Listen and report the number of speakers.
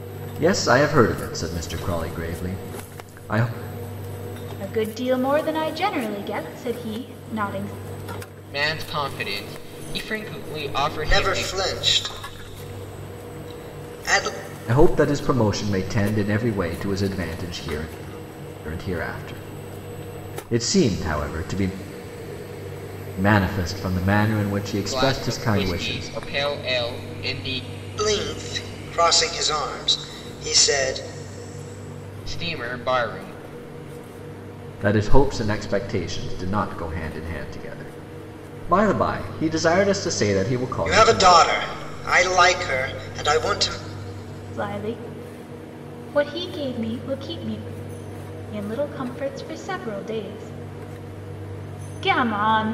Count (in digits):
4